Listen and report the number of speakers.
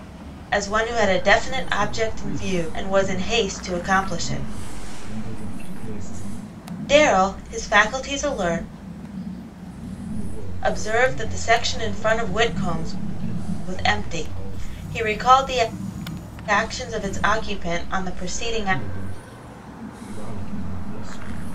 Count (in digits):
2